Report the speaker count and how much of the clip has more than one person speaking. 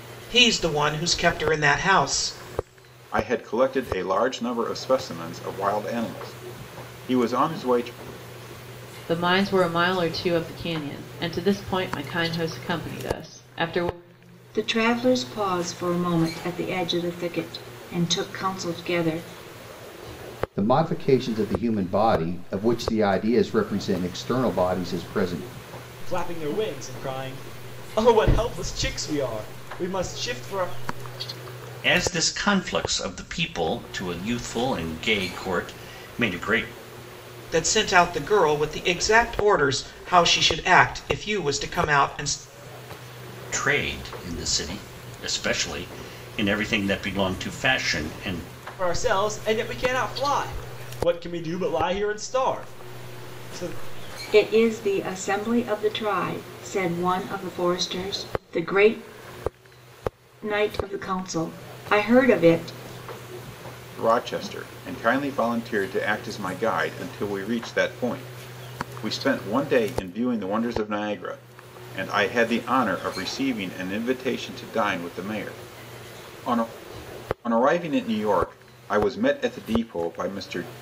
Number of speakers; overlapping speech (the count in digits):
7, no overlap